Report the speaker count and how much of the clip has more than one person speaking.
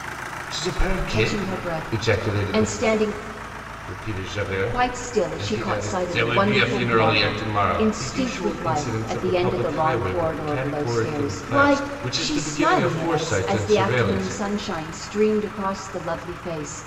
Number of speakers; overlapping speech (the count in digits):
2, about 69%